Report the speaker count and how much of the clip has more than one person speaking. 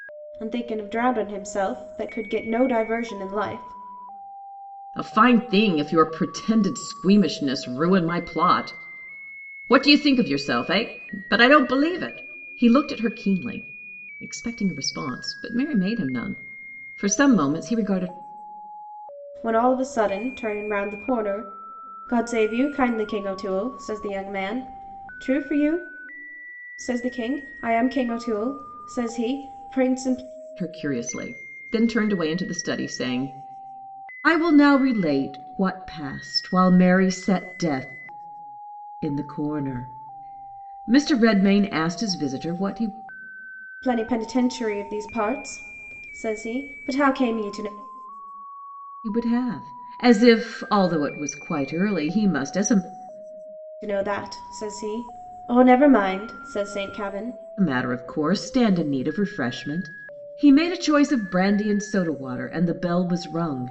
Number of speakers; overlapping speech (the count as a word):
two, no overlap